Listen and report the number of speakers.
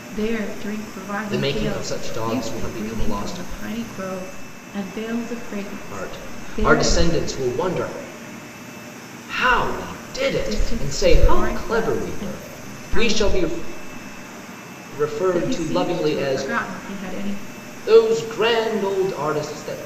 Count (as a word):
two